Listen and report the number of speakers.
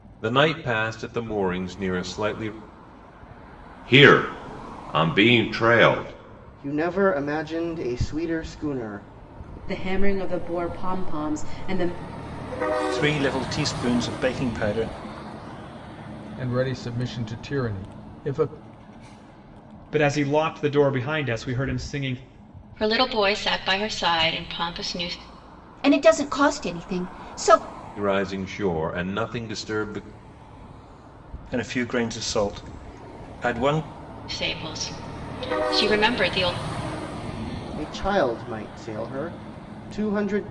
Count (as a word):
nine